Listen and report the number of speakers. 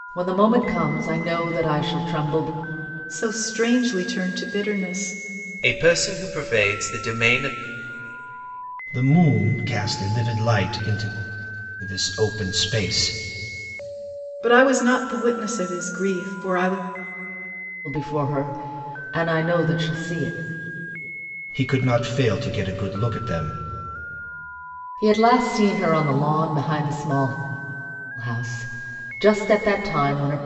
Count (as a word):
four